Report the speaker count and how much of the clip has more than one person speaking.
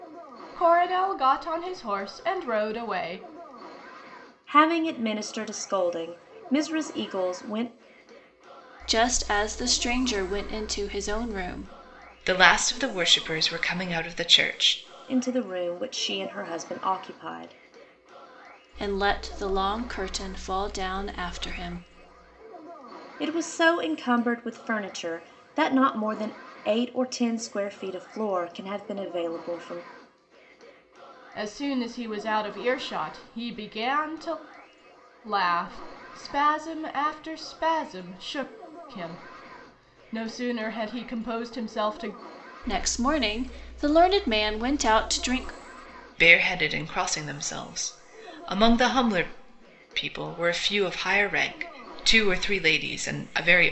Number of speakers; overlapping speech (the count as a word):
four, no overlap